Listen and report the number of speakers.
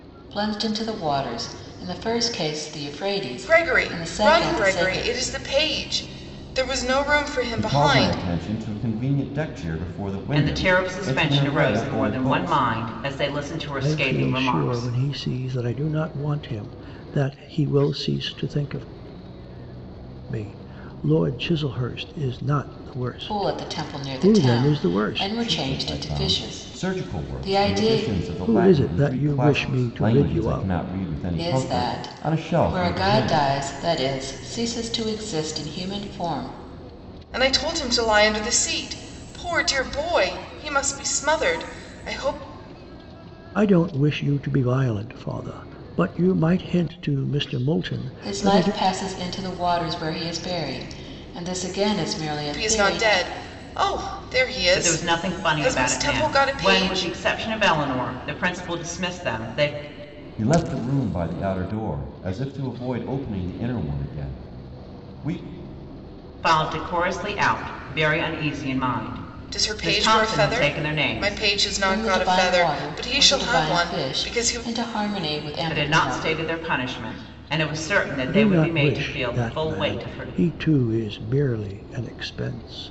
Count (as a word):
five